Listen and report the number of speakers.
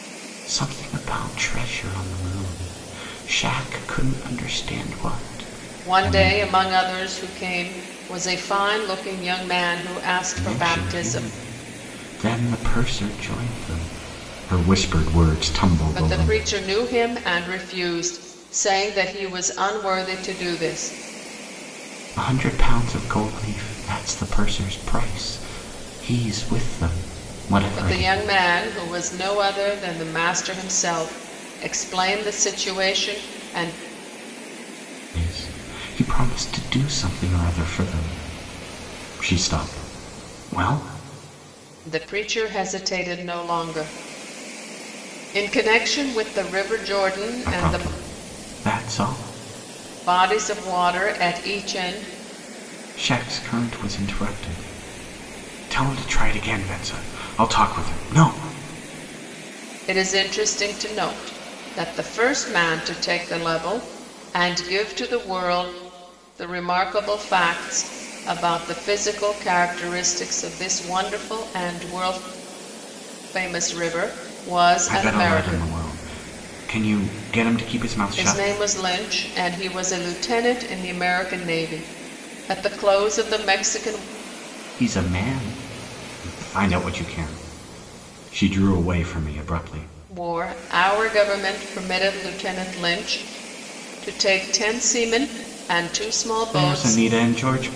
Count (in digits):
2